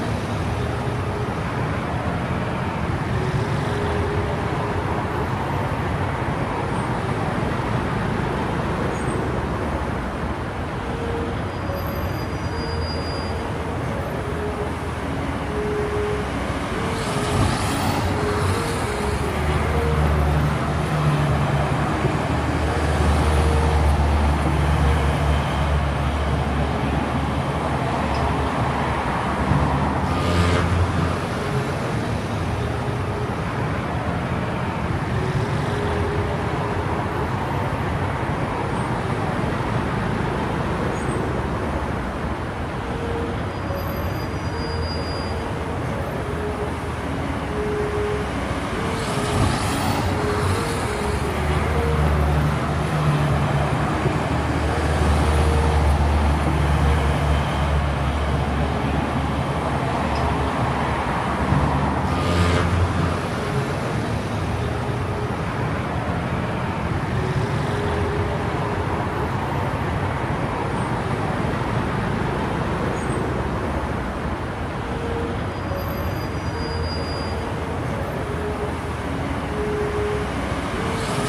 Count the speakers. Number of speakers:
zero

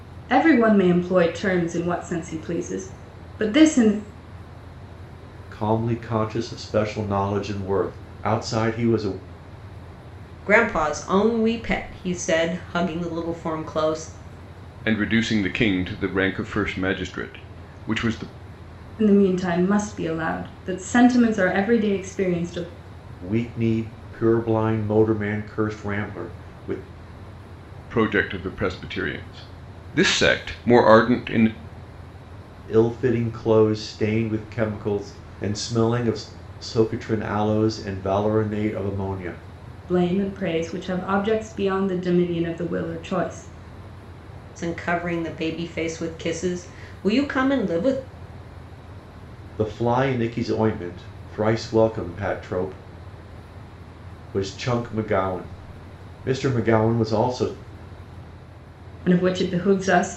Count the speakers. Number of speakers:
four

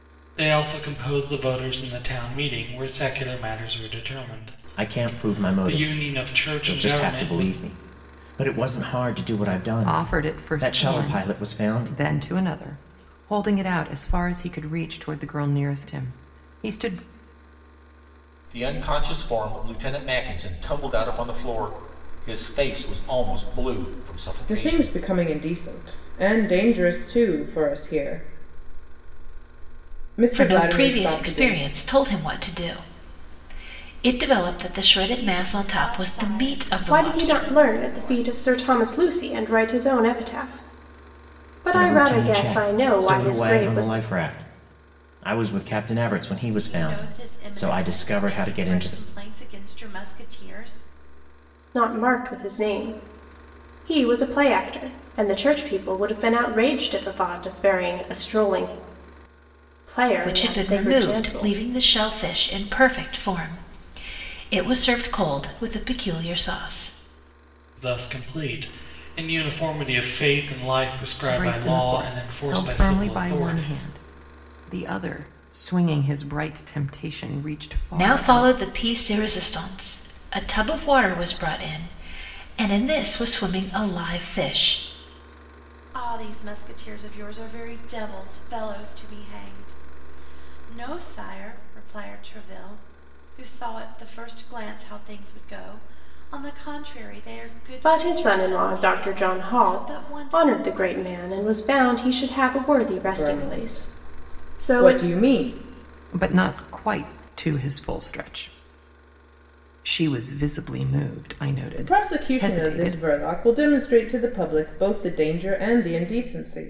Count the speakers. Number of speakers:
eight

